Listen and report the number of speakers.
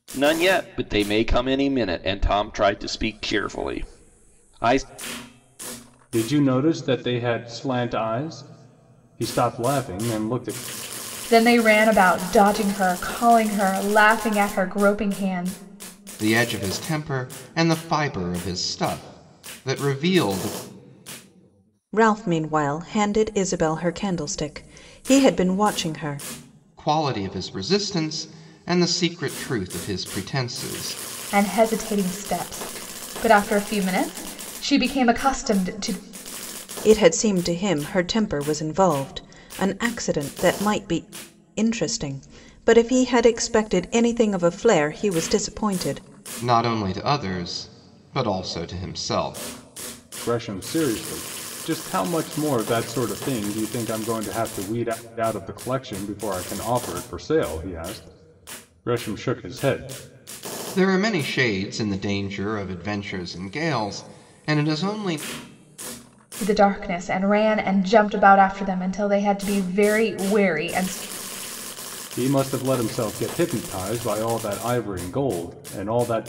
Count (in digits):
5